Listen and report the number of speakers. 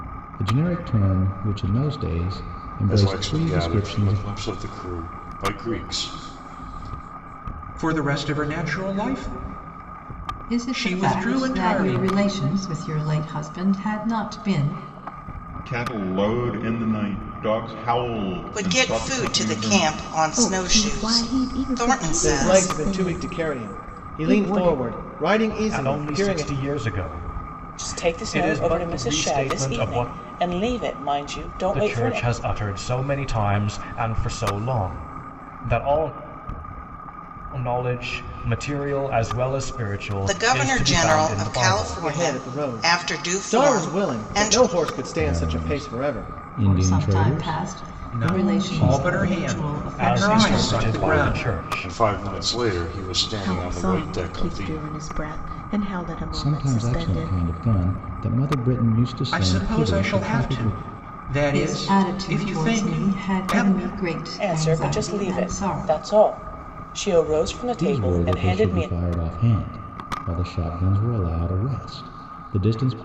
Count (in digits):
10